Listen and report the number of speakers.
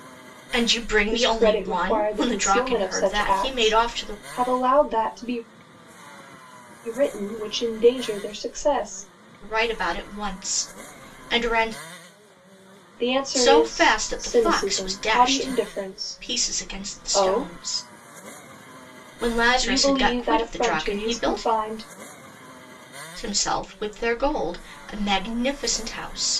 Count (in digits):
2